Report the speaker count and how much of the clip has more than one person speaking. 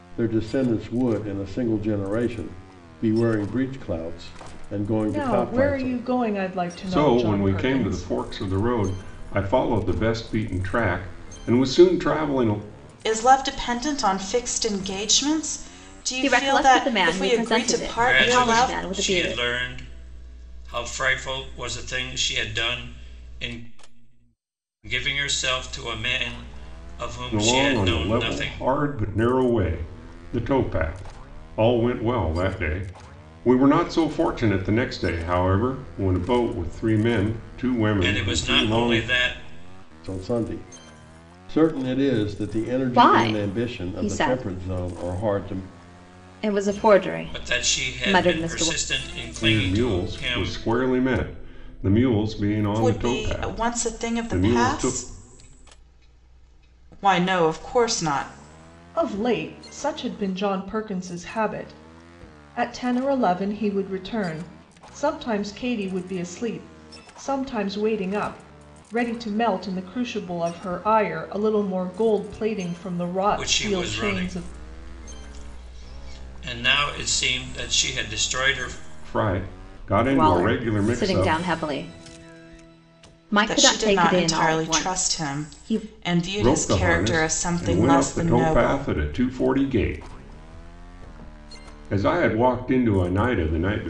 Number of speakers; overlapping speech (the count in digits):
6, about 25%